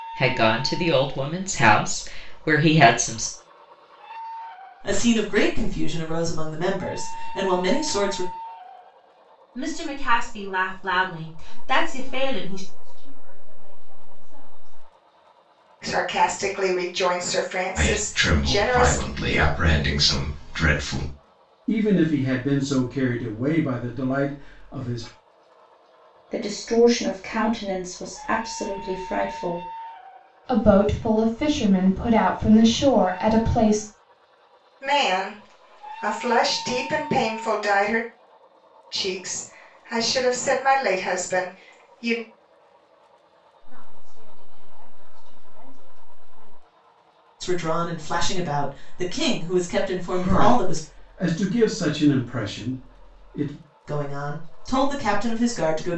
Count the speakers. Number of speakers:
nine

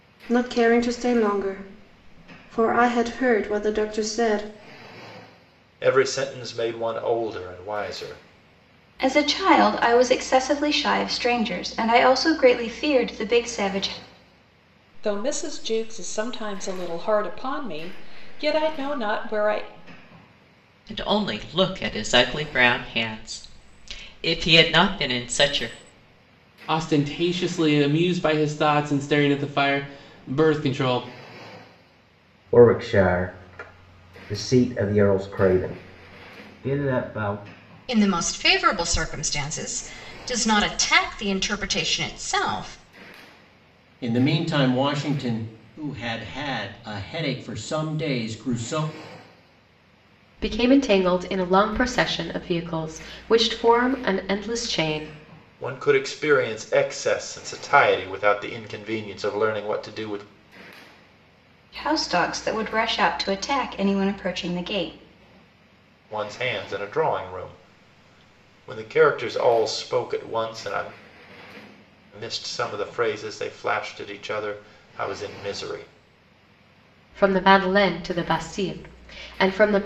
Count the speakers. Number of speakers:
ten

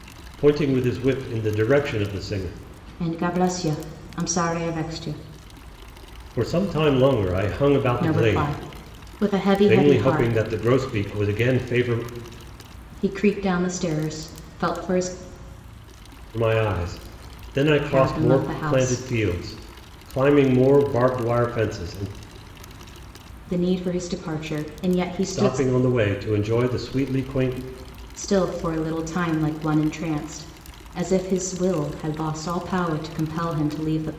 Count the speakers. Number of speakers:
two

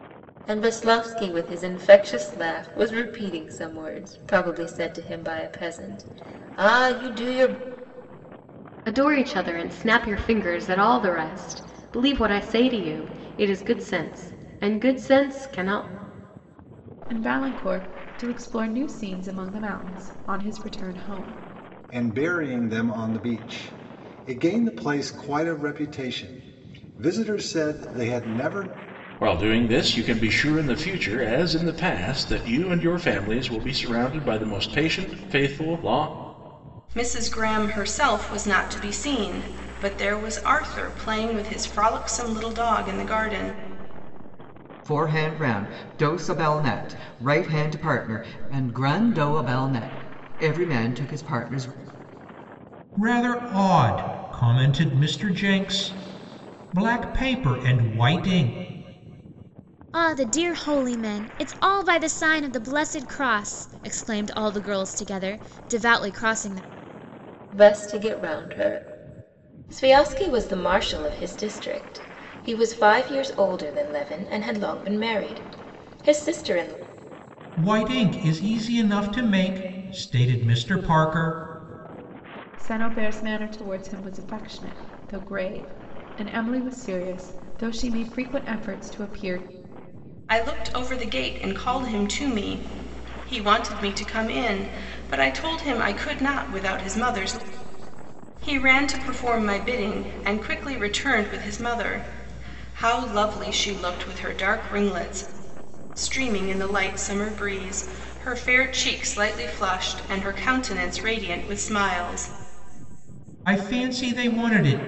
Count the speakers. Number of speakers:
nine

